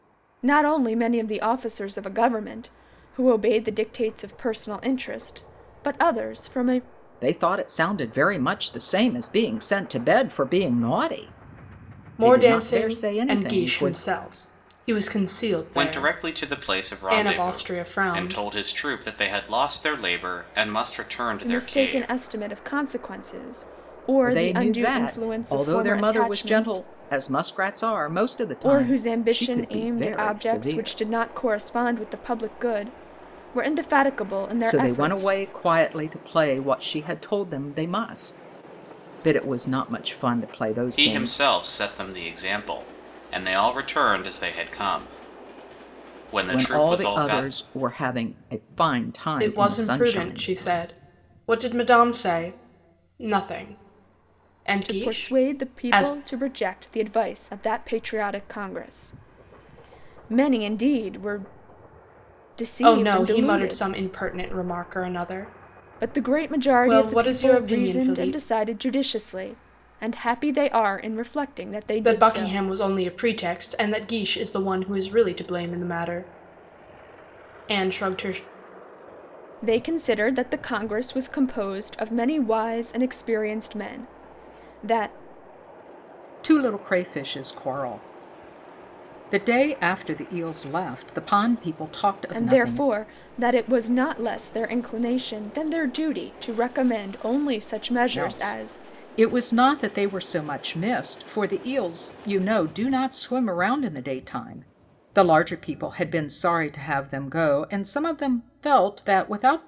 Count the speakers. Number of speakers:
4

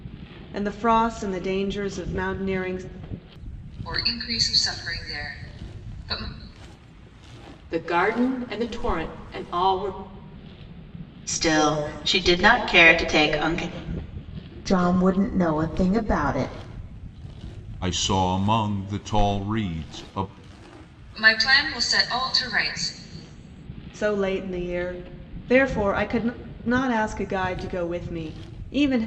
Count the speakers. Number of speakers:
6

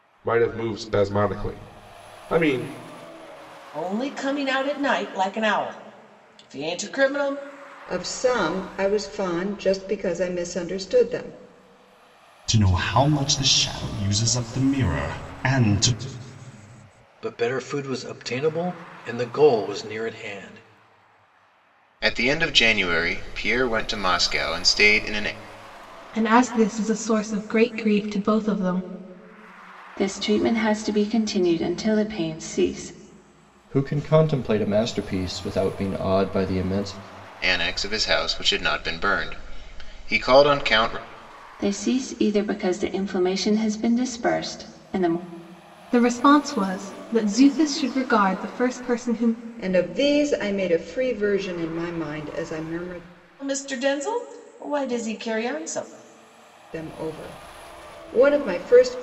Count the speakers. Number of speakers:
9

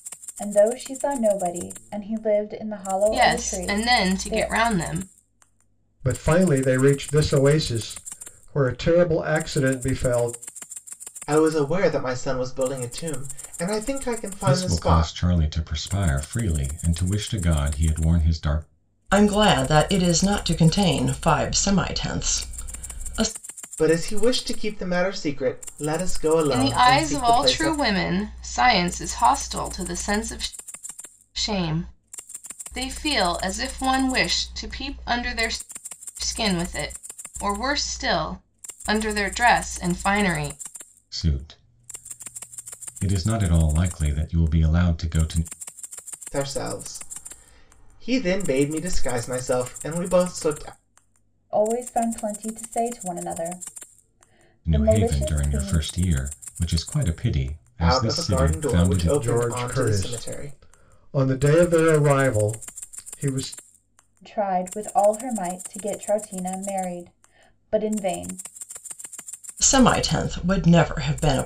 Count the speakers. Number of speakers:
6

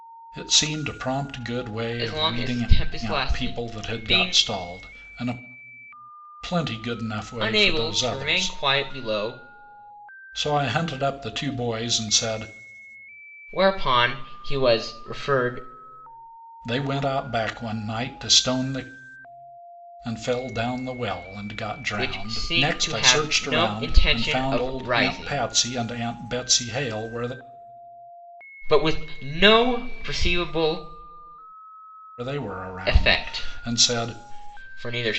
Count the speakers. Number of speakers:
2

